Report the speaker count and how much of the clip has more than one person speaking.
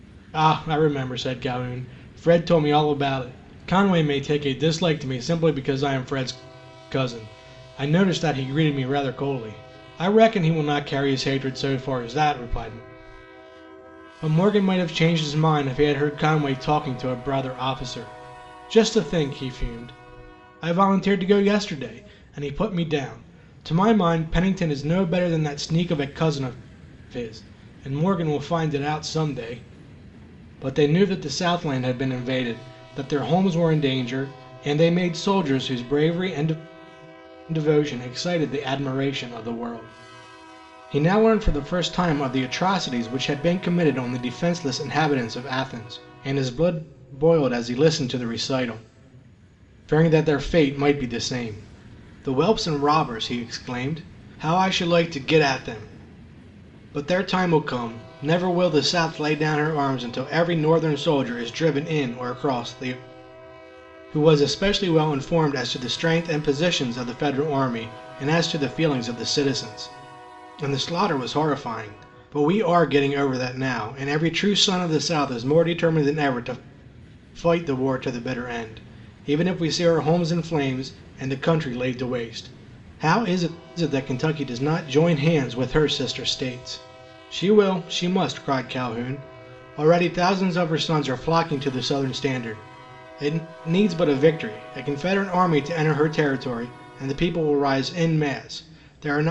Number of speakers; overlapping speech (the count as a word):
one, no overlap